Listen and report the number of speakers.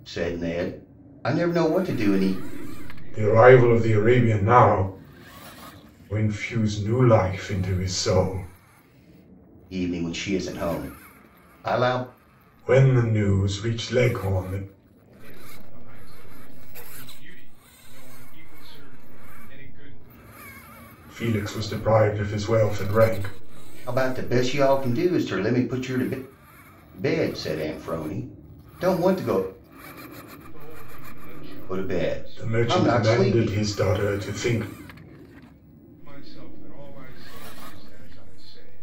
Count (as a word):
three